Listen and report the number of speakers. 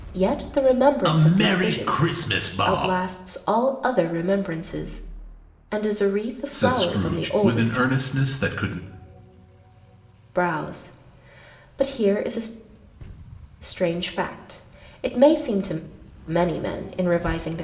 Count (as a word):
two